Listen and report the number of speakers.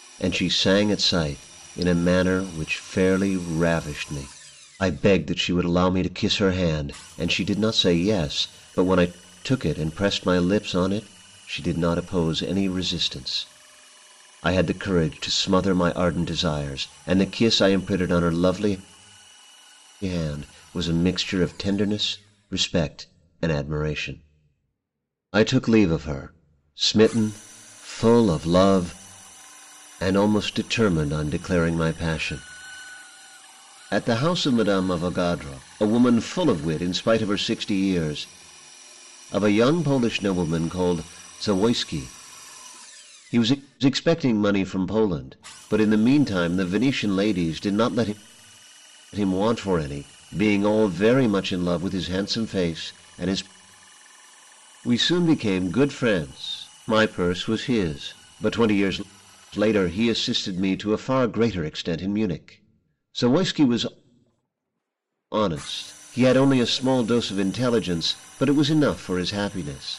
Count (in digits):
1